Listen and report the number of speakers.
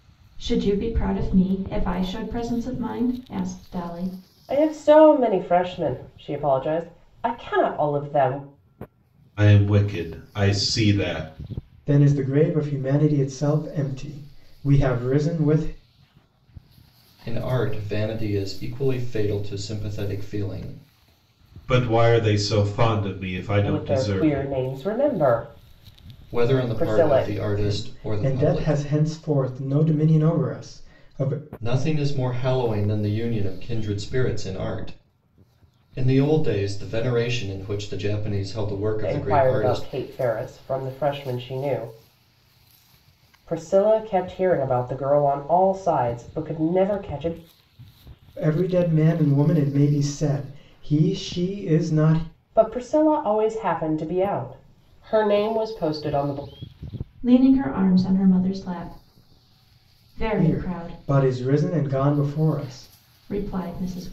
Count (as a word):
five